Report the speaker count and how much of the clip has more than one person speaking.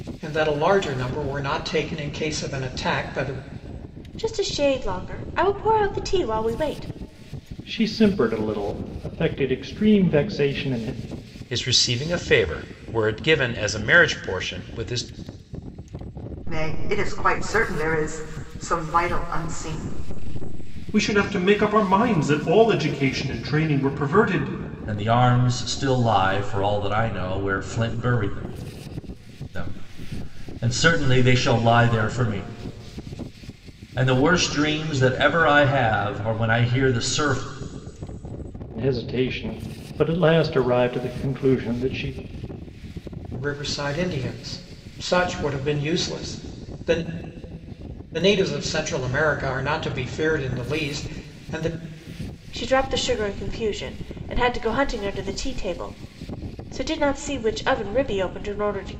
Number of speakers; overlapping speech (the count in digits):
7, no overlap